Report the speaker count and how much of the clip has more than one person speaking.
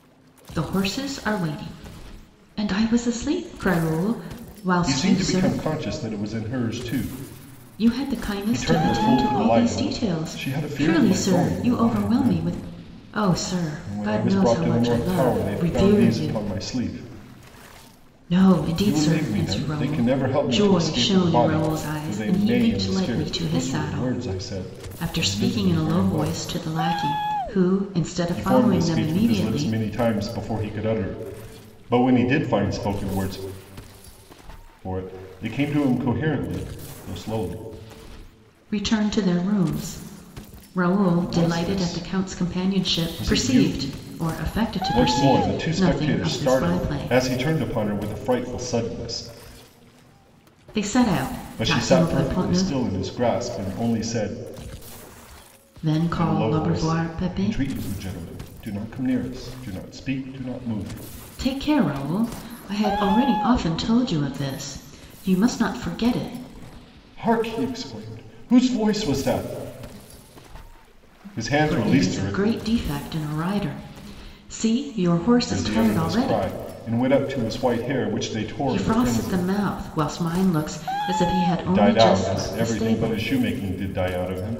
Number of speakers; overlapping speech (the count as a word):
two, about 34%